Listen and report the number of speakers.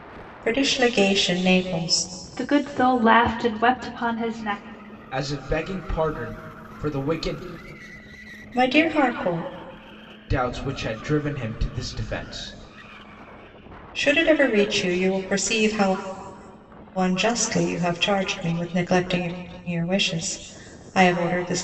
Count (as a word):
three